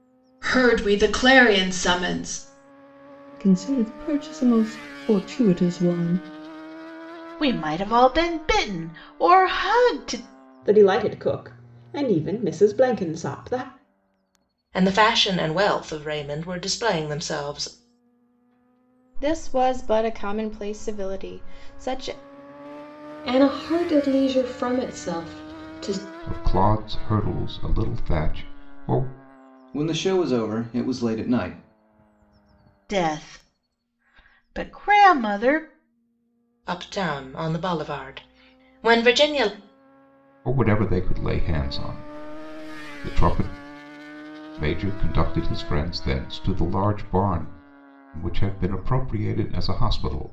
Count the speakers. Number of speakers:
nine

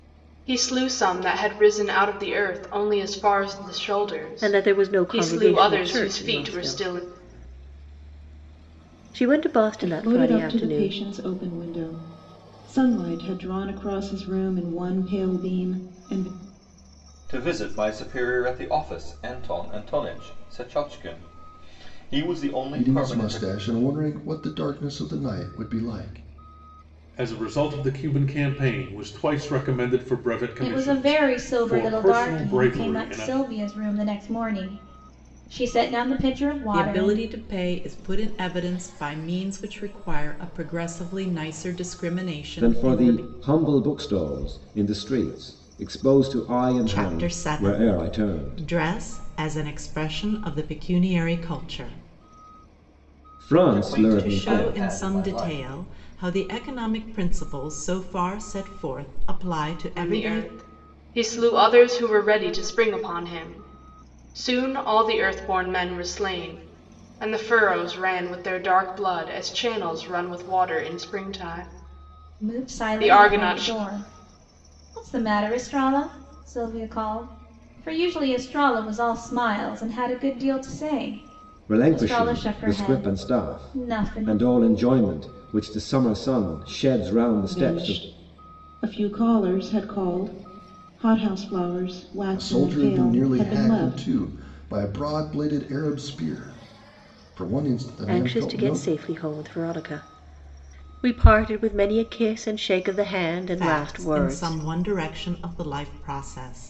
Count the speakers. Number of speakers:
nine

